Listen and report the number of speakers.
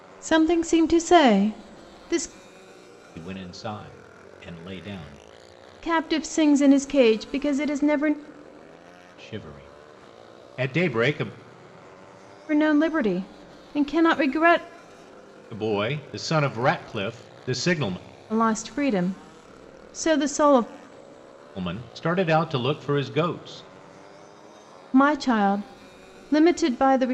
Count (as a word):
two